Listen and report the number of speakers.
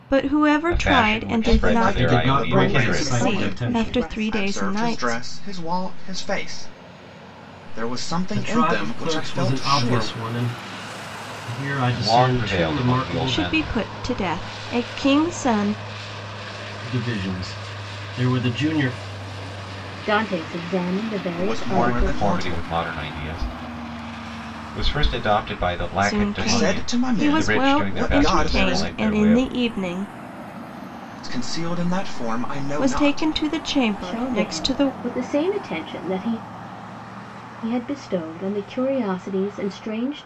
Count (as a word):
five